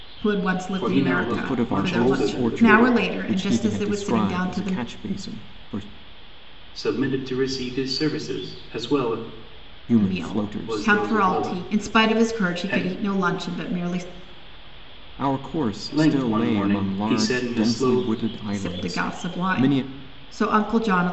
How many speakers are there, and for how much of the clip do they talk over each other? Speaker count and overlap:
three, about 50%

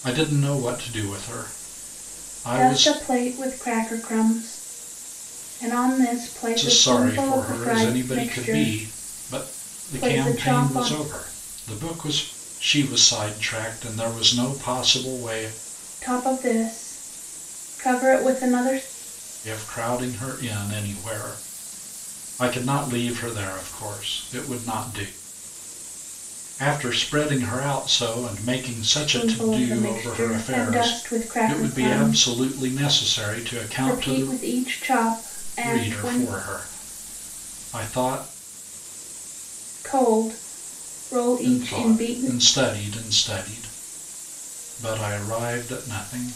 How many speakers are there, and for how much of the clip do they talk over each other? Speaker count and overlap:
two, about 21%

